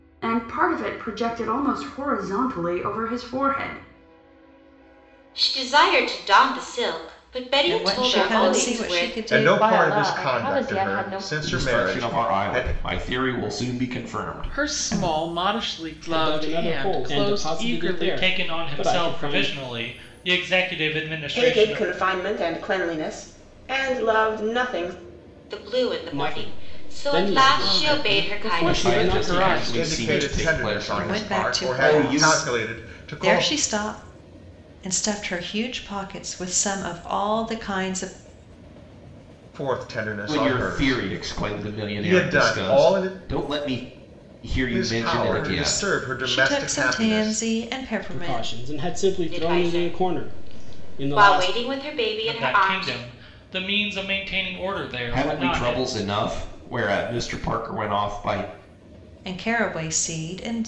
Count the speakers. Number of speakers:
ten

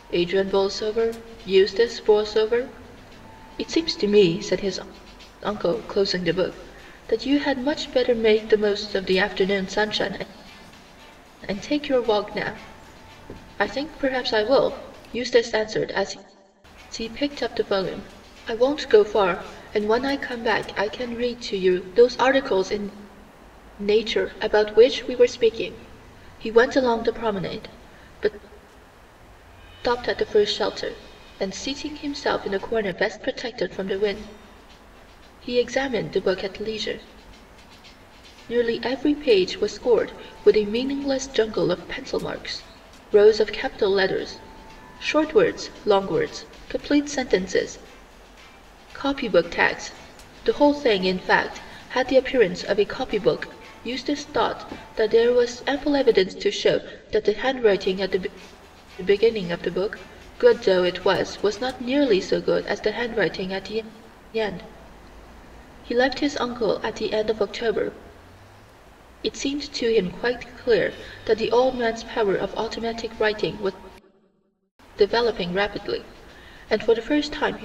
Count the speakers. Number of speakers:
one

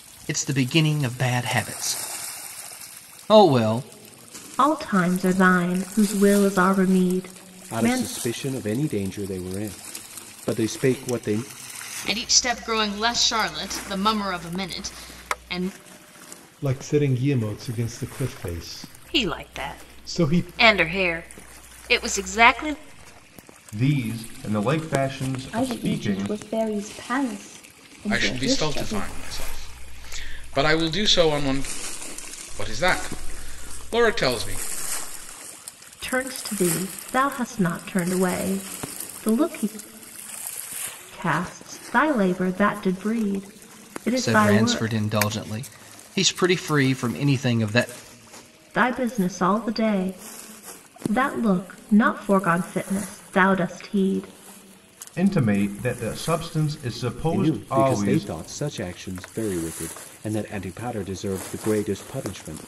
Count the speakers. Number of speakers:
nine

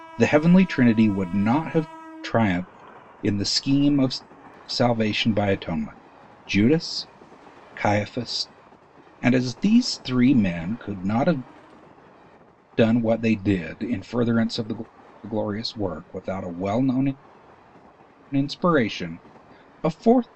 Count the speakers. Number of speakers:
one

